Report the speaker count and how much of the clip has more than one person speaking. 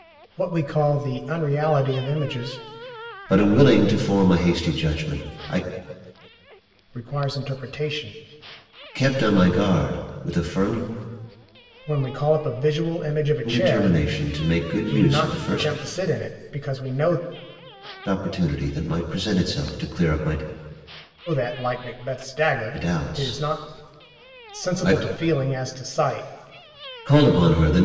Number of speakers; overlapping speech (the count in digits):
2, about 10%